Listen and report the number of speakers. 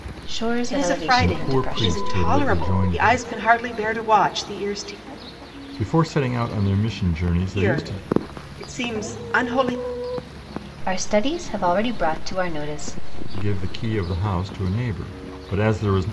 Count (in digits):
3